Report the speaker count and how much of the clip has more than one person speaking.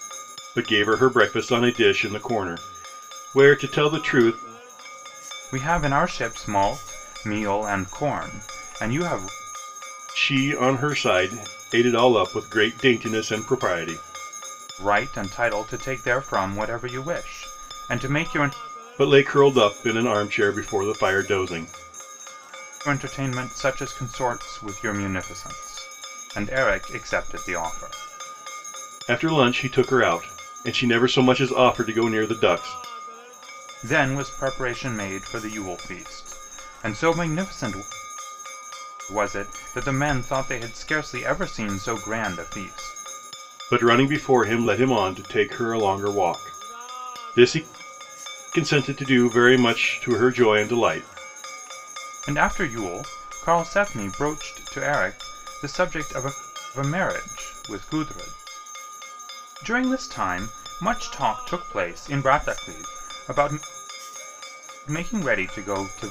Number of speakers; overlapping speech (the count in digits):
2, no overlap